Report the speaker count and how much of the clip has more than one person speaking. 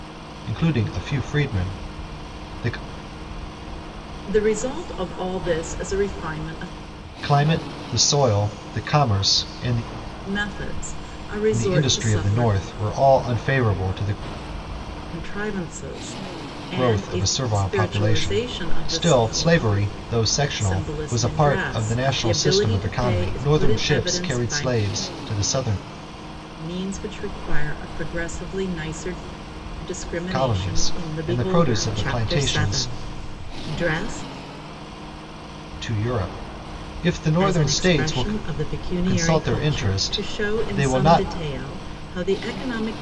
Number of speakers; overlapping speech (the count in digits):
2, about 32%